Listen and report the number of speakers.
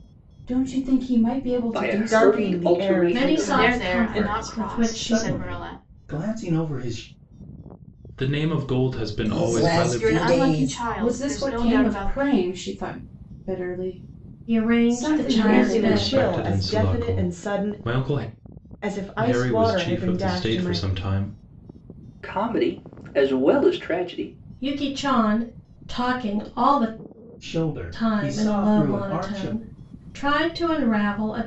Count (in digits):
8